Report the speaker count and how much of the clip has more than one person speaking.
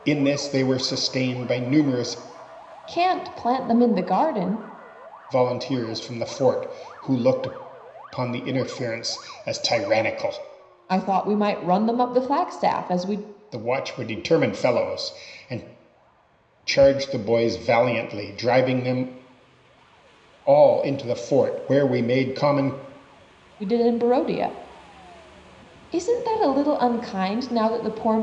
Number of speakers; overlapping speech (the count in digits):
2, no overlap